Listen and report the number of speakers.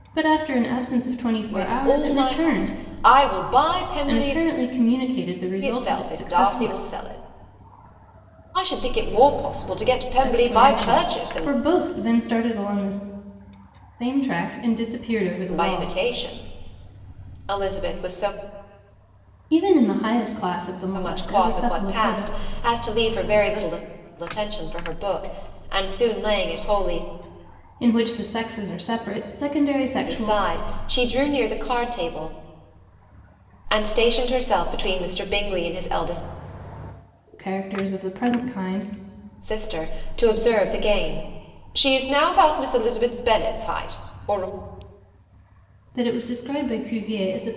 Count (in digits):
2